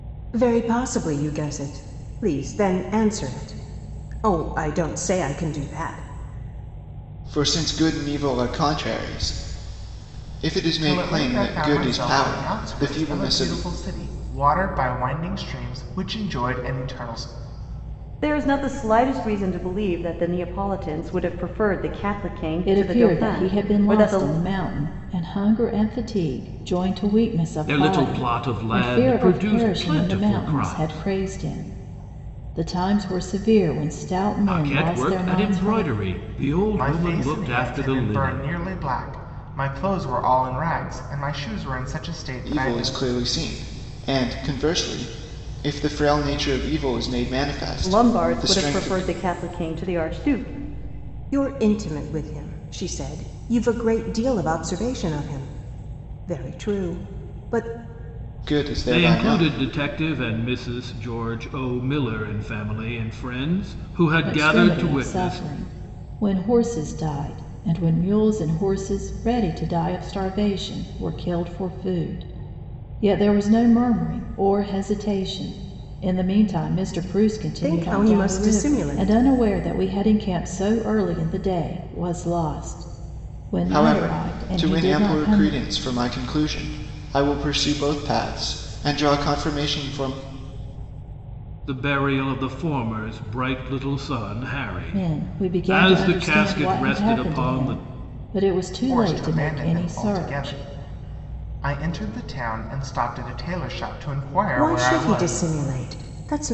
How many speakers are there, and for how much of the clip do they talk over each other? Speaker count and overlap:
6, about 23%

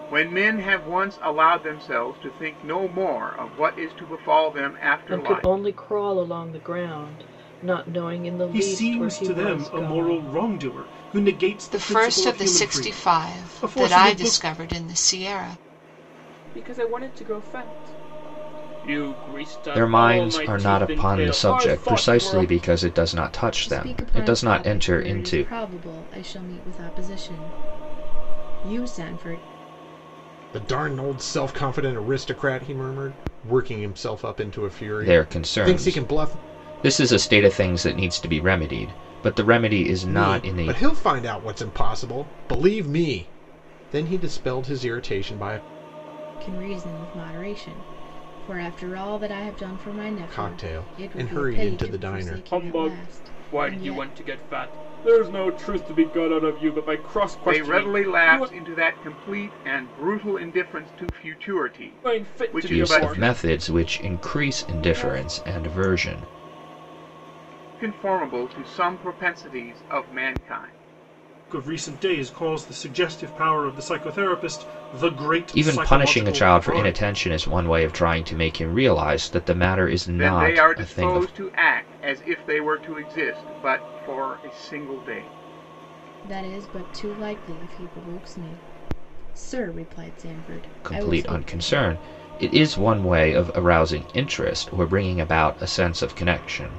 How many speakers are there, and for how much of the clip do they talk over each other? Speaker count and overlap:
8, about 25%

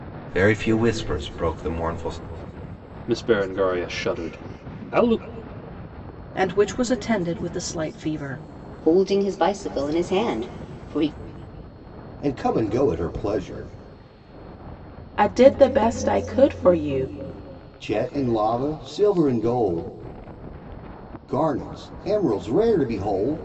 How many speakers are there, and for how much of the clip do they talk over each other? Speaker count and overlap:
6, no overlap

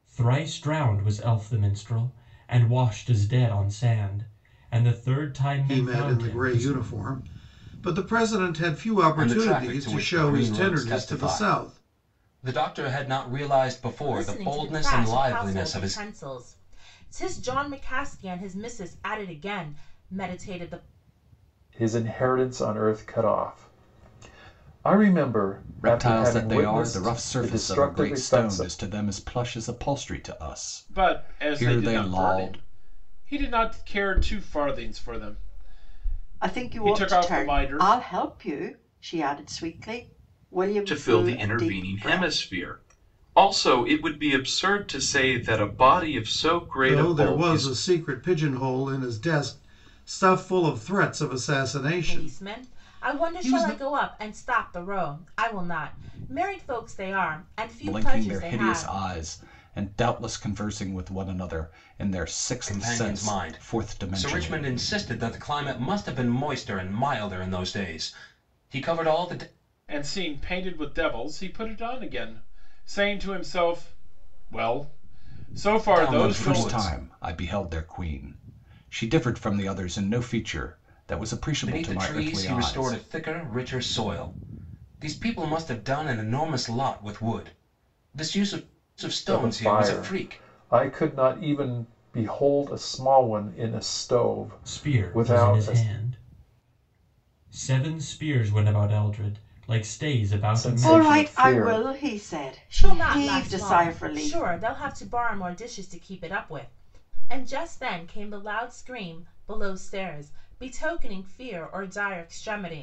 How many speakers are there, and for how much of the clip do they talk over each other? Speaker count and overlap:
9, about 24%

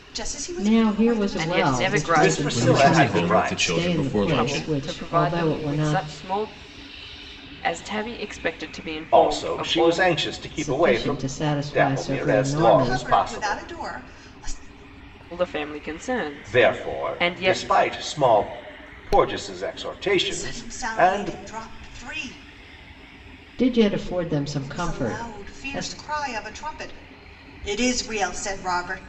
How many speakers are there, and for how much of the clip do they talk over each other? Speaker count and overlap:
5, about 44%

